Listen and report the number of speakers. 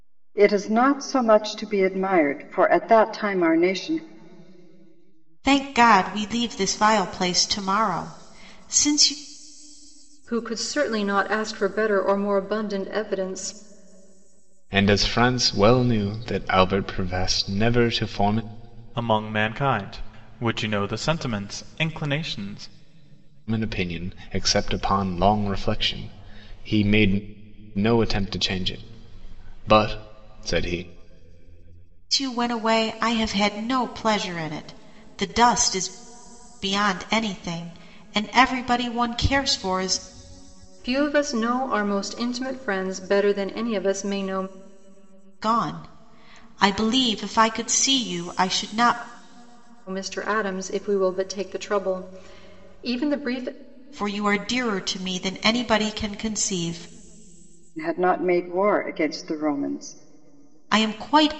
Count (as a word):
five